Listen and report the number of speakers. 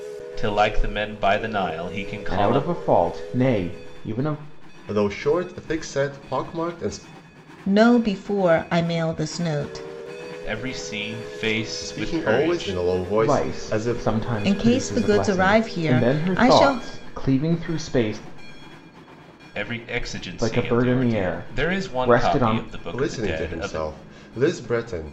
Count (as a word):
four